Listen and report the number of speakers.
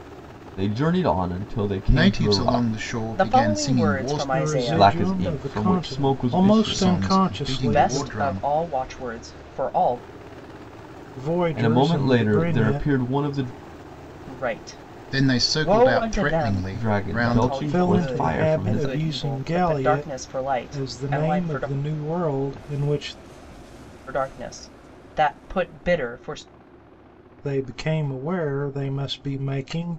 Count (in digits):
4